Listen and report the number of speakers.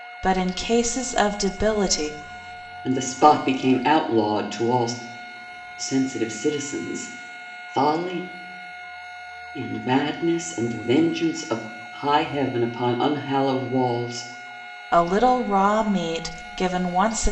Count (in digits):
2